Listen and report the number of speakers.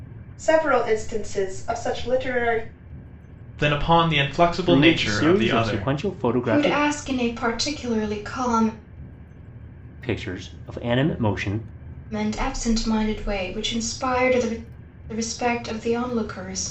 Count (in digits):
4